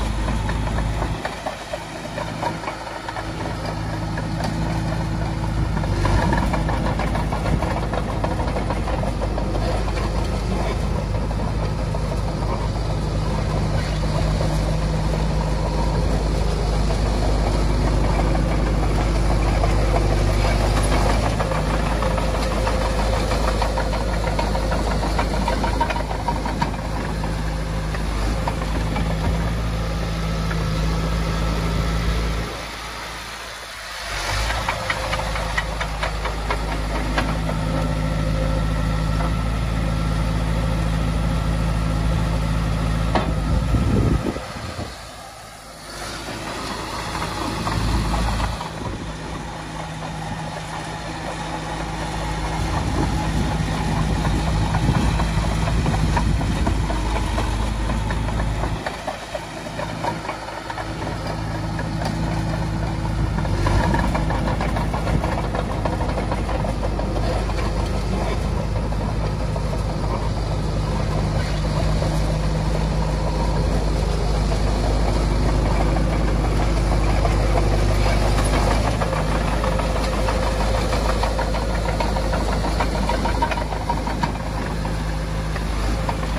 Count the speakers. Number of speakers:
0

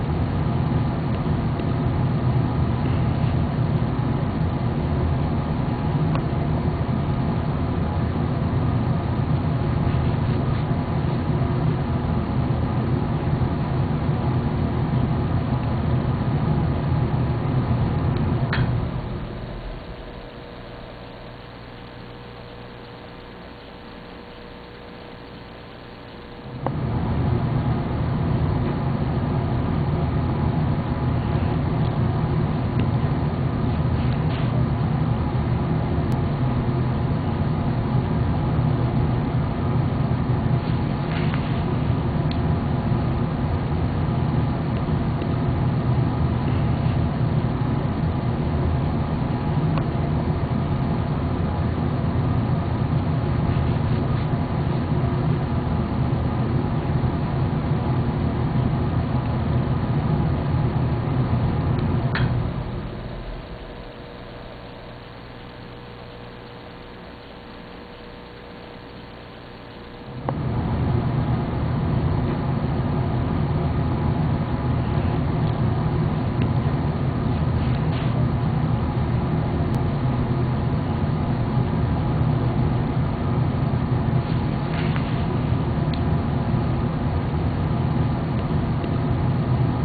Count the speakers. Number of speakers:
0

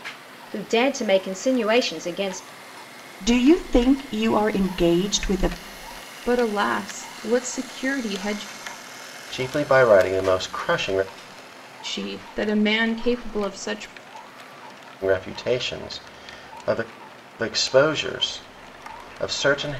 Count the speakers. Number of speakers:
4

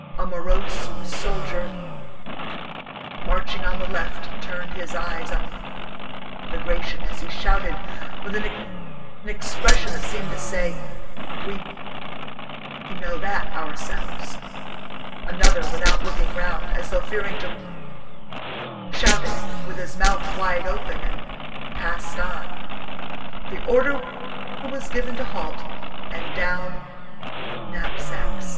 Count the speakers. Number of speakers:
1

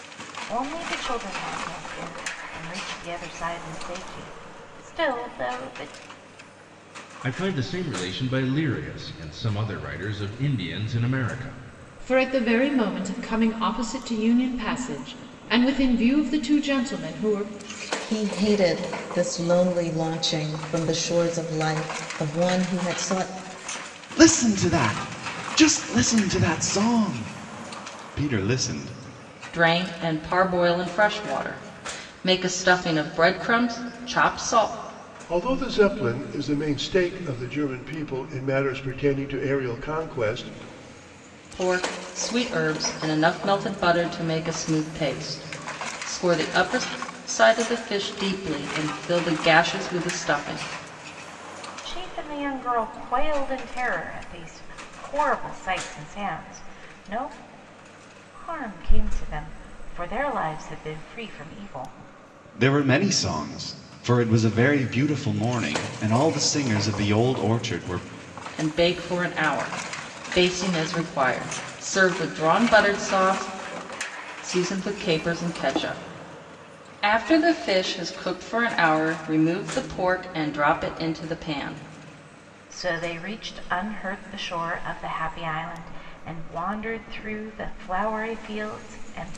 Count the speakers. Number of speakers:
7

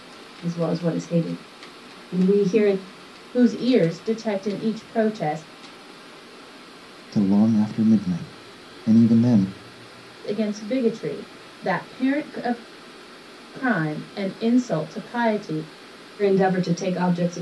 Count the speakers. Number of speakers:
3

